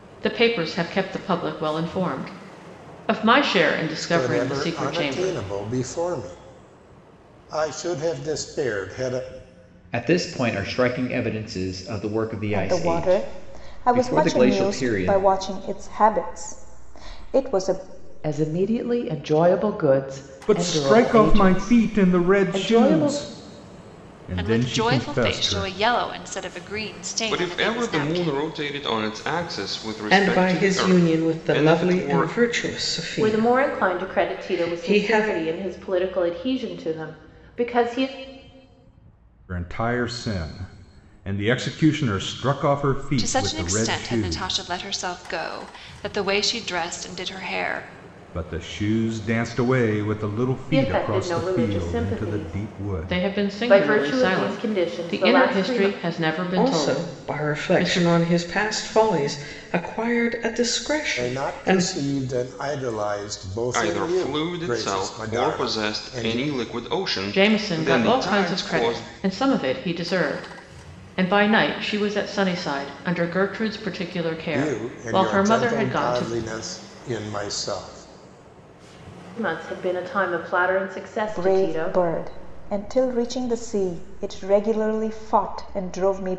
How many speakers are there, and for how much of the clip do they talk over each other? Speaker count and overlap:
ten, about 35%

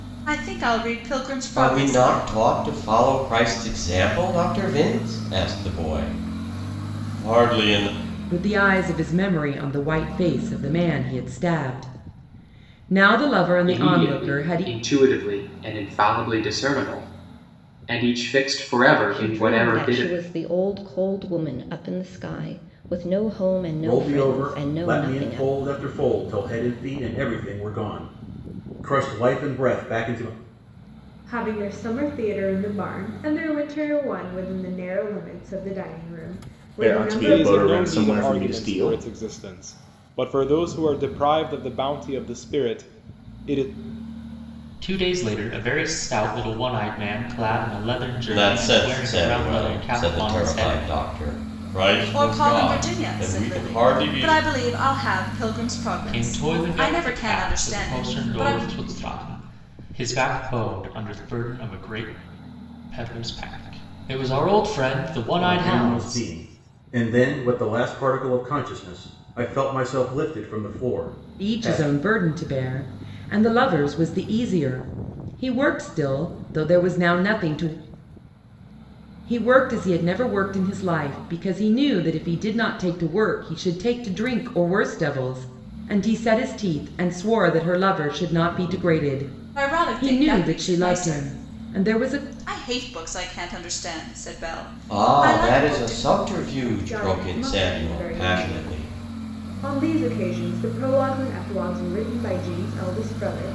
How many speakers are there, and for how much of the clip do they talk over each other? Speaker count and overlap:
ten, about 21%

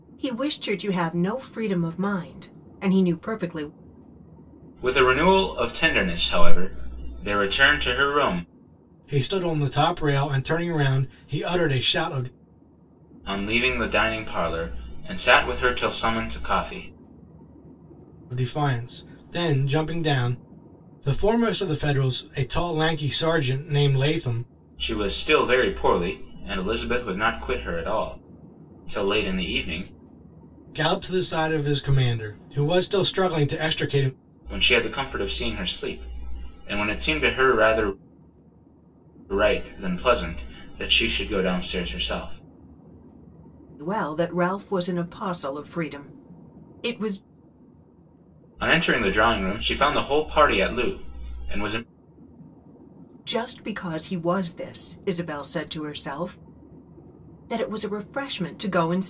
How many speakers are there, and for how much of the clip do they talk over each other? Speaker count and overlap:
three, no overlap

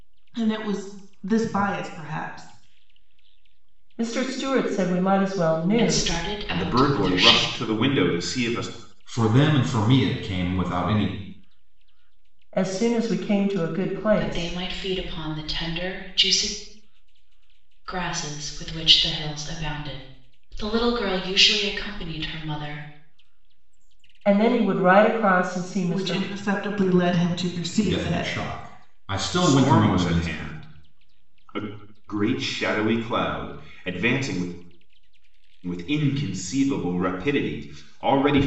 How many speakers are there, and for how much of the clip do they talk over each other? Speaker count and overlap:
five, about 10%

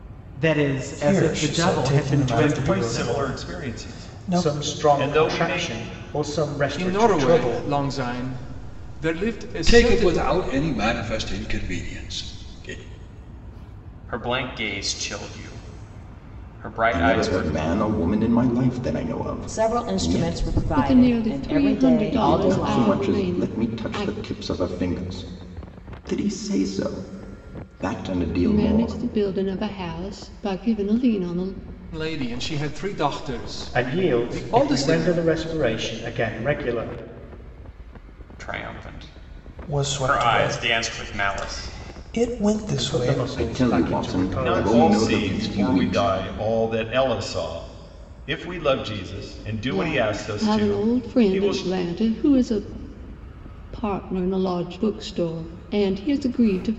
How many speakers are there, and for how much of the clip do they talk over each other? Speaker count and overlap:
ten, about 37%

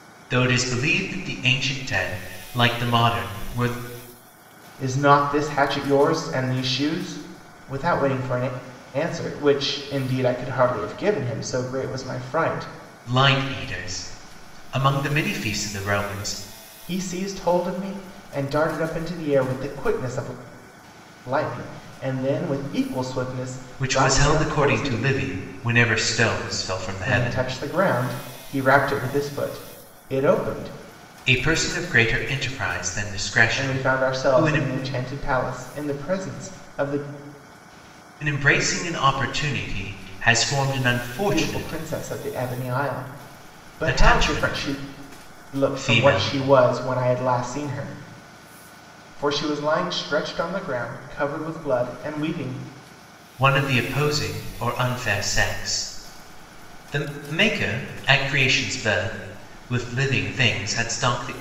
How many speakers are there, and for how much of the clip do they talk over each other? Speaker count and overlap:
two, about 9%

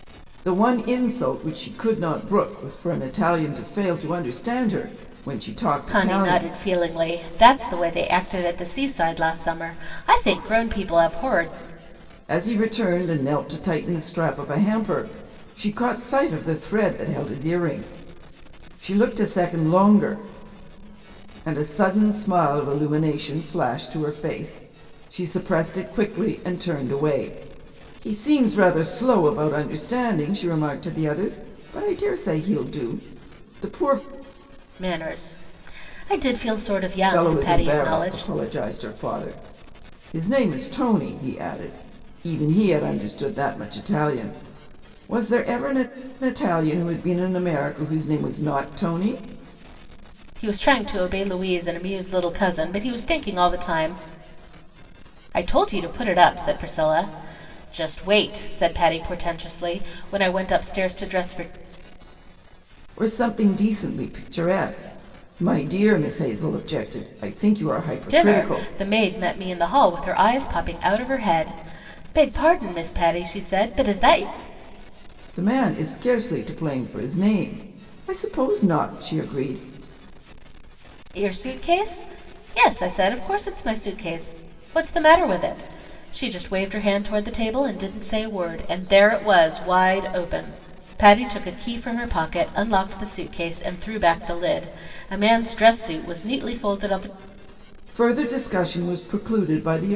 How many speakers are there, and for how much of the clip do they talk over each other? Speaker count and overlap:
two, about 3%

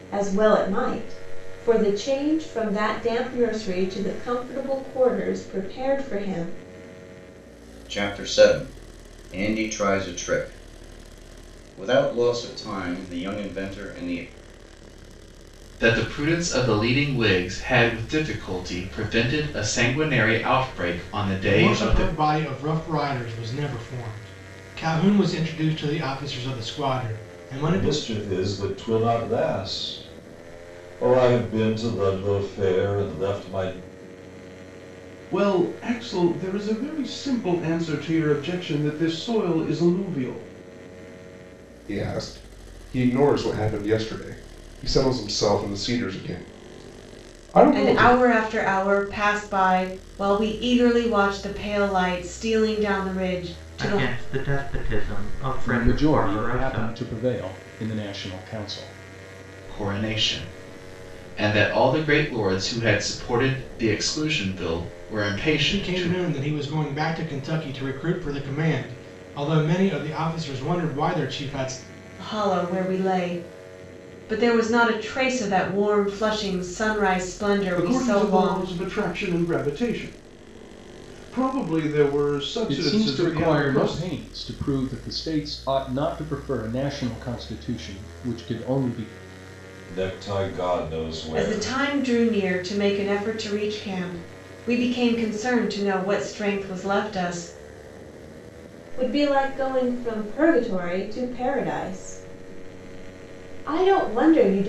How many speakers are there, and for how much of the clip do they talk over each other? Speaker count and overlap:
ten, about 6%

